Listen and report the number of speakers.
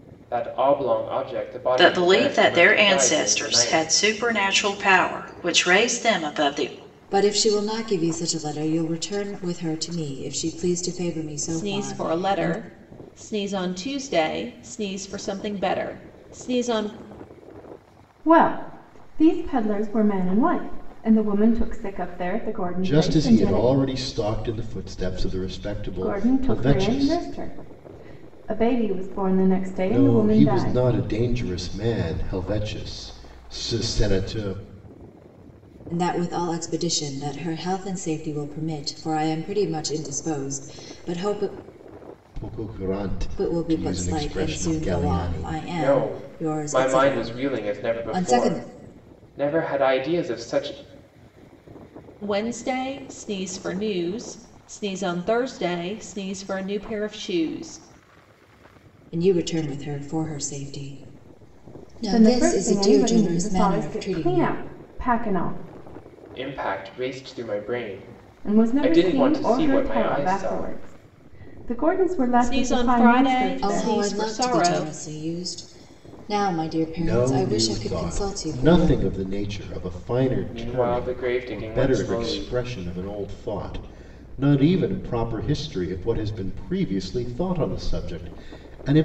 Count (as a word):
six